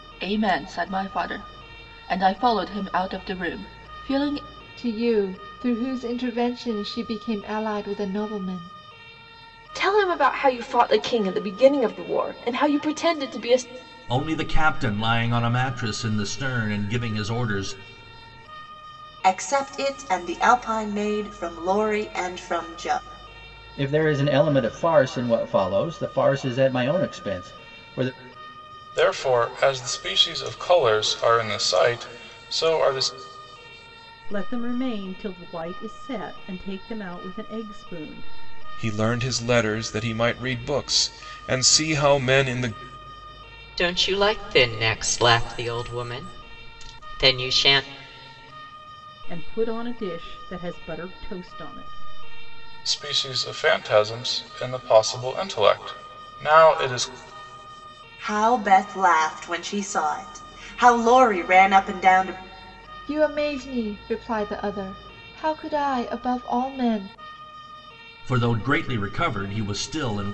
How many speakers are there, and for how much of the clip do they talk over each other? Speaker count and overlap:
10, no overlap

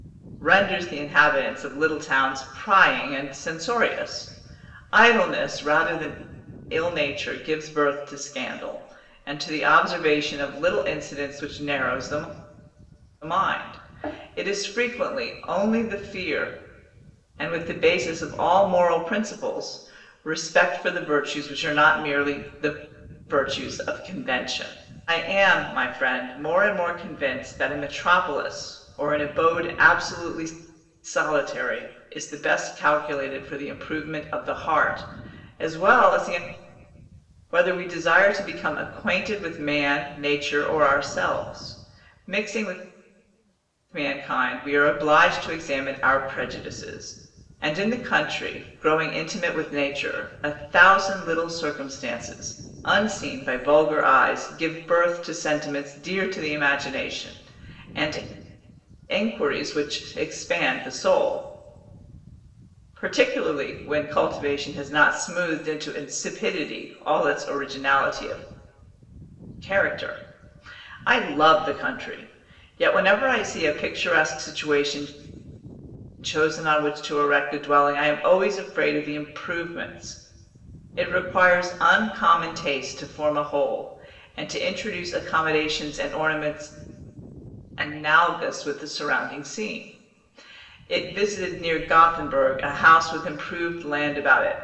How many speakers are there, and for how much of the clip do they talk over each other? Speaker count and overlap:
1, no overlap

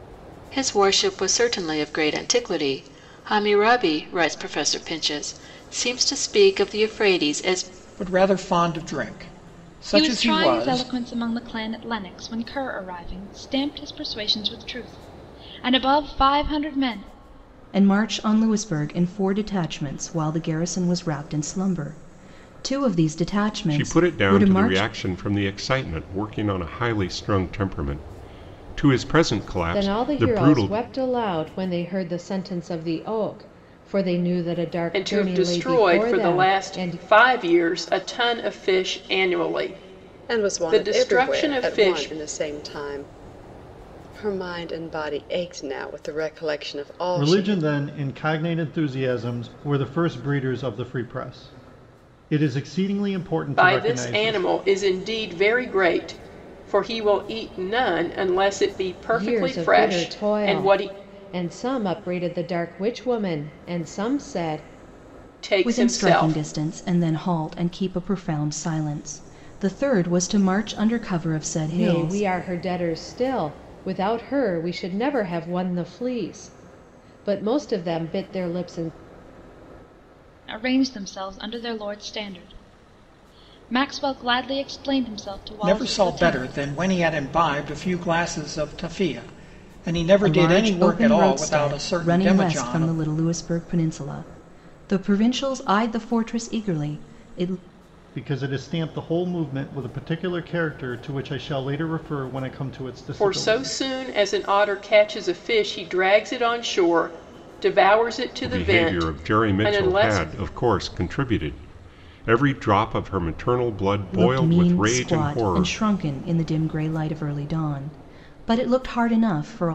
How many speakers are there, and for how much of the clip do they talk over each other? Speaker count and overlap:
9, about 17%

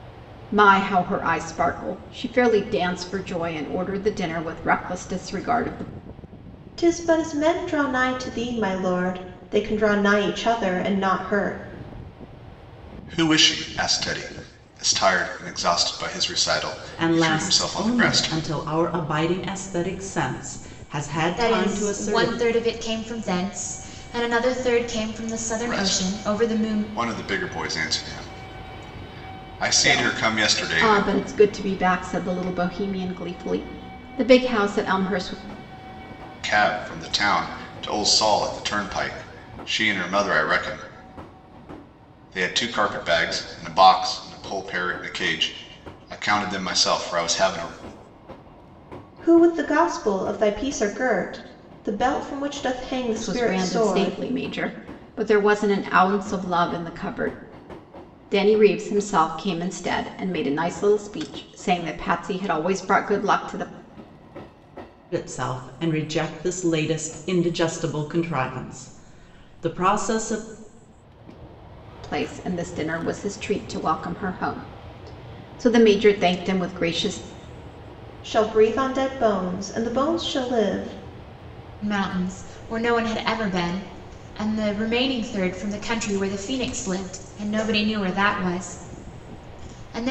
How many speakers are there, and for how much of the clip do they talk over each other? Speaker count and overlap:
5, about 7%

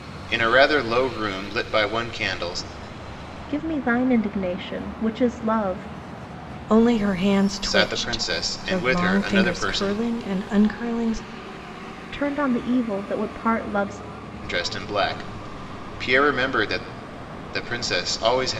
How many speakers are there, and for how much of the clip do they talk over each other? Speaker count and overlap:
3, about 13%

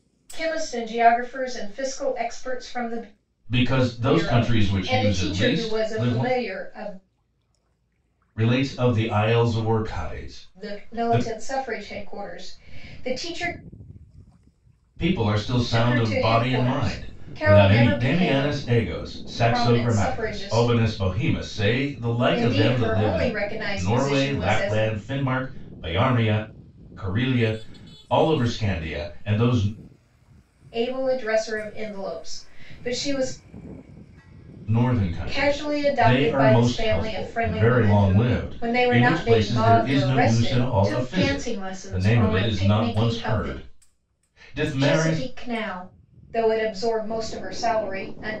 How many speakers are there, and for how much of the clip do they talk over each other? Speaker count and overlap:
2, about 37%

